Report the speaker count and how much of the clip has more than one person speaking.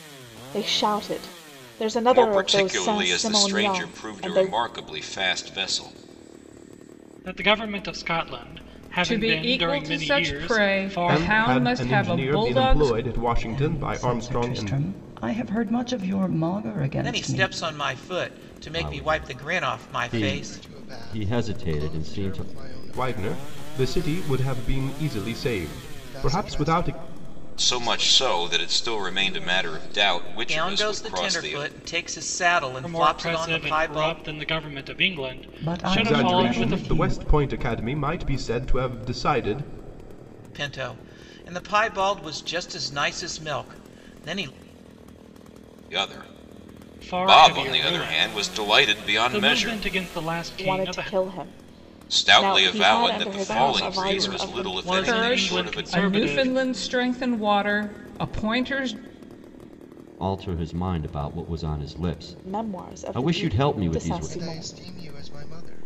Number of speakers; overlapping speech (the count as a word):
nine, about 48%